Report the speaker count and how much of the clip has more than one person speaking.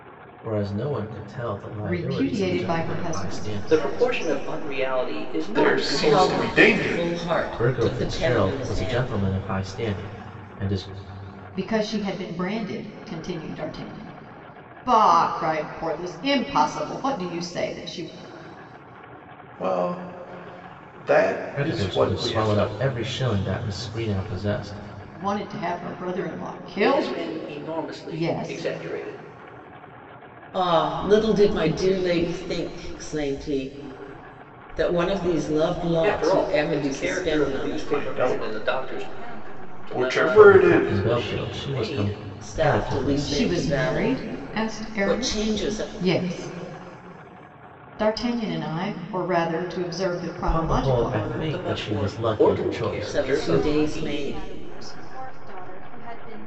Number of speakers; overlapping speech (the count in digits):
6, about 43%